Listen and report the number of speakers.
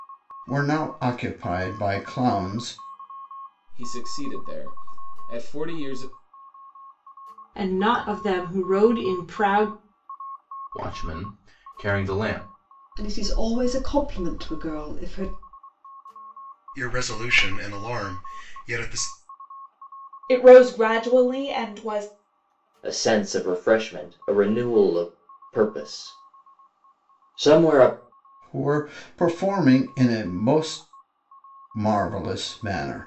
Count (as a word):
eight